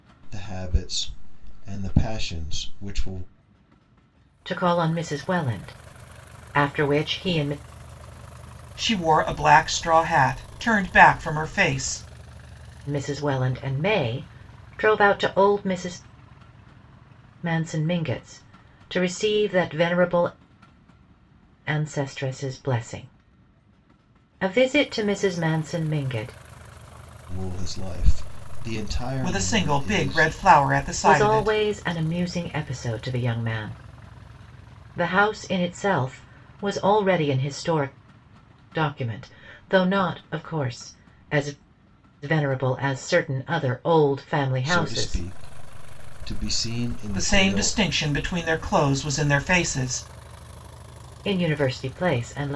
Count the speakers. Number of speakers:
3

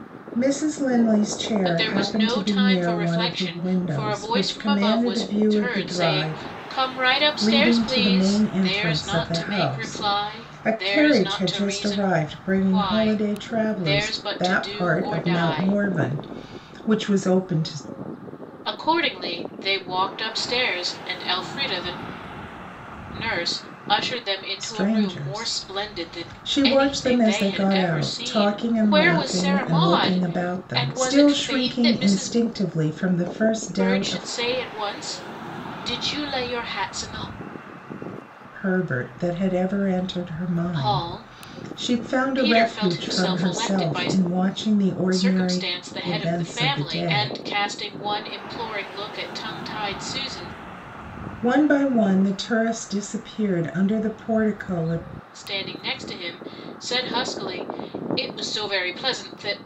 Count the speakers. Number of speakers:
2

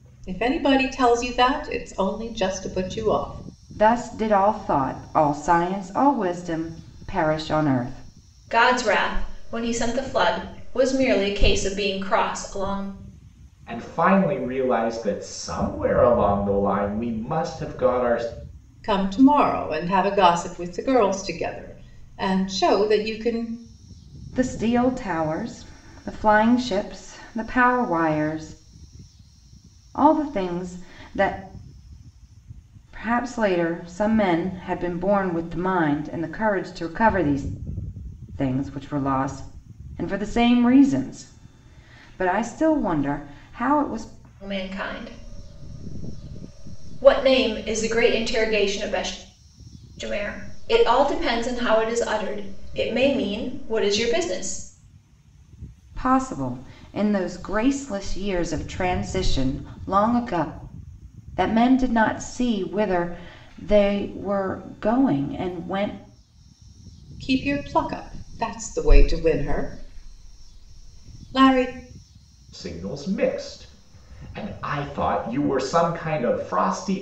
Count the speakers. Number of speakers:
4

